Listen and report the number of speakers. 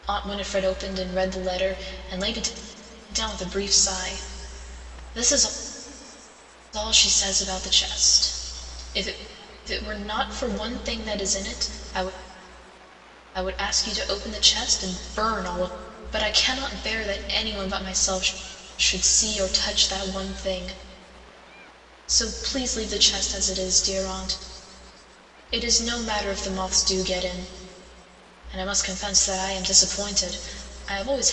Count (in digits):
1